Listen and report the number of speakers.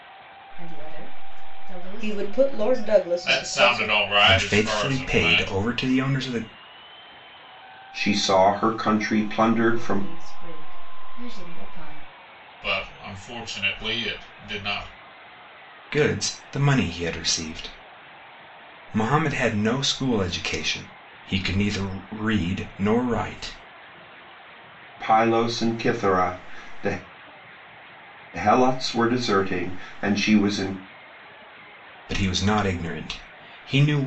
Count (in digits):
5